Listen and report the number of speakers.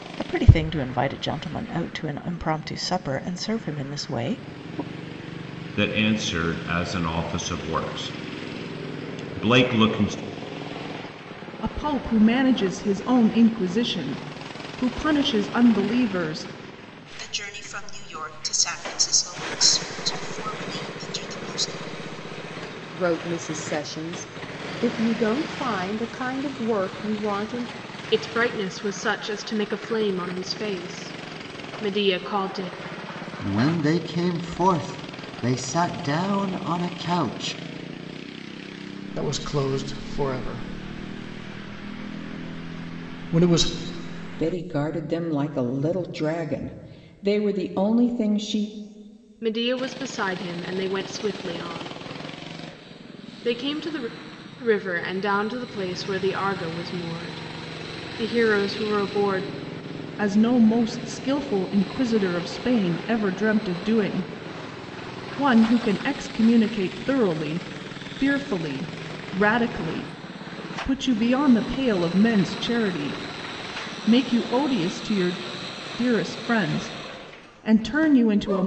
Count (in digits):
9